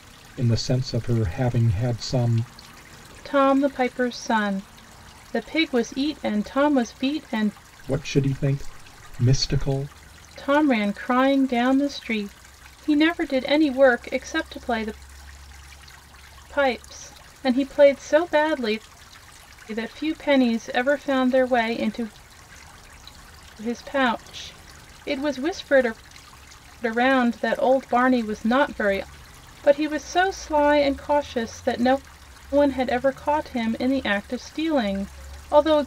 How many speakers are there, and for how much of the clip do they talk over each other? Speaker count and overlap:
2, no overlap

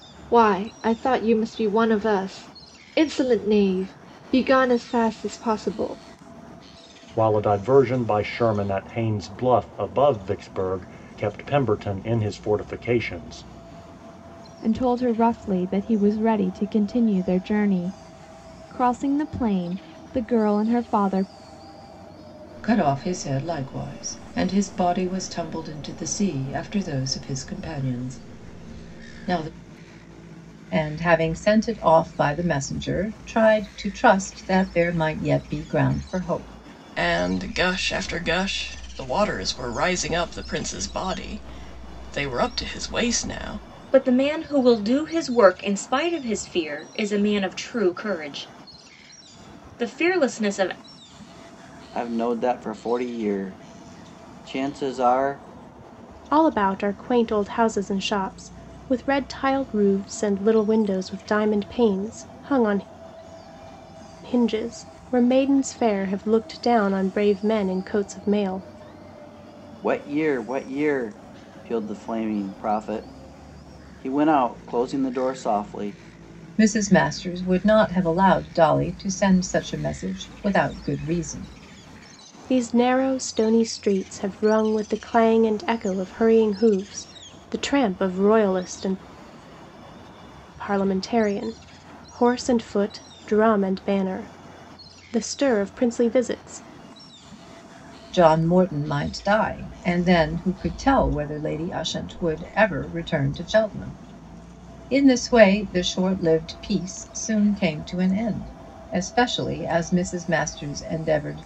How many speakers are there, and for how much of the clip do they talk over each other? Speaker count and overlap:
9, no overlap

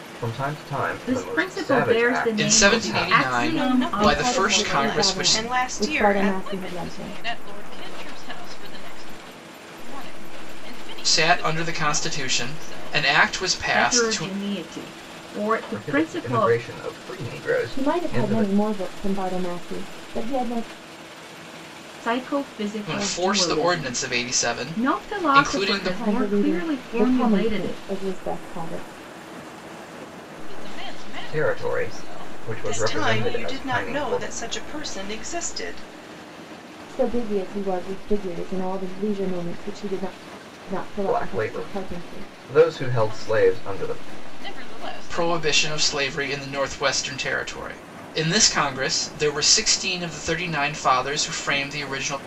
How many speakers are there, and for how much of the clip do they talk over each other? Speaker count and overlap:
6, about 43%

